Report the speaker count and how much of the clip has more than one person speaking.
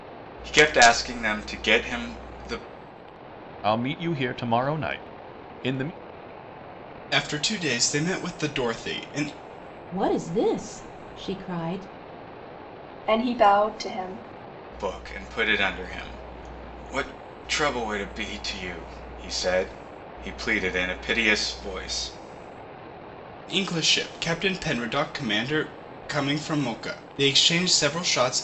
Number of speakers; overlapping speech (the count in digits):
5, no overlap